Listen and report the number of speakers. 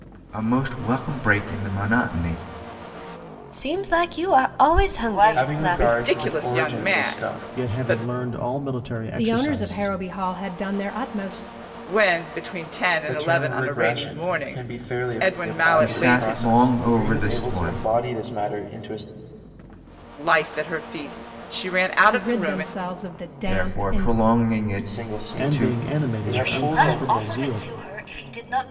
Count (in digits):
7